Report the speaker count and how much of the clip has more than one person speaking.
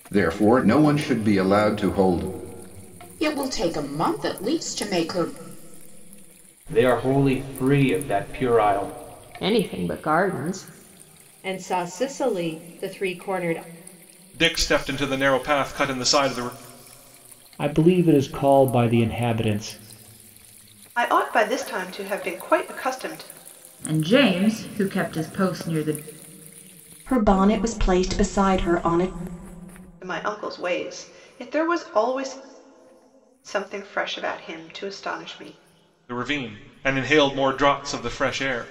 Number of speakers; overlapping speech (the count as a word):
ten, no overlap